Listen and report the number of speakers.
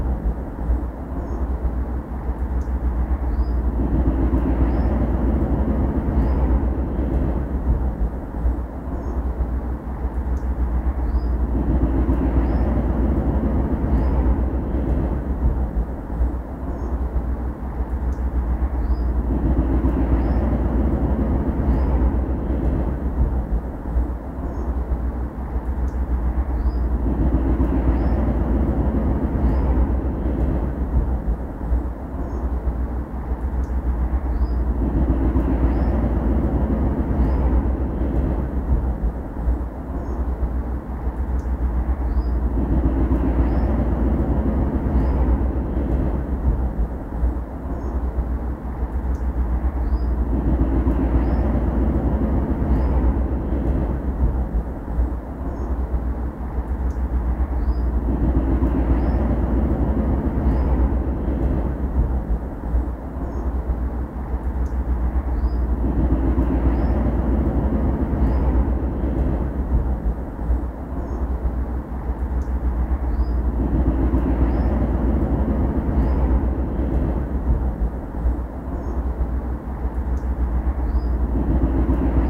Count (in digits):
0